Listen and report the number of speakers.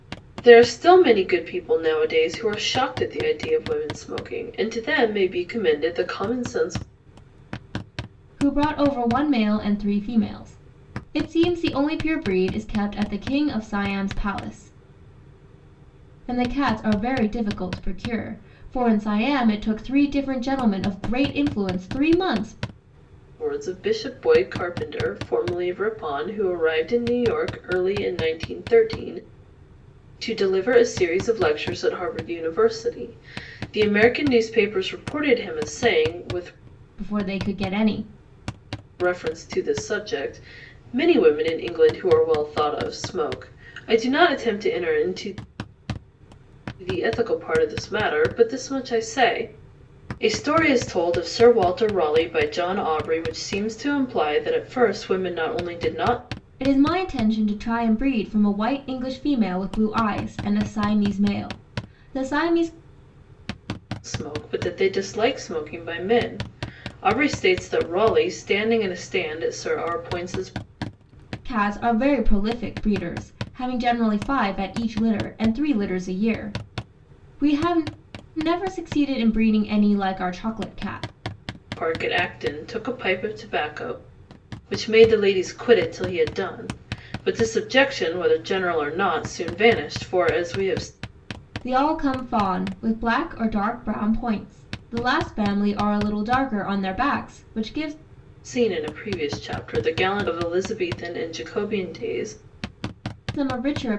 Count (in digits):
2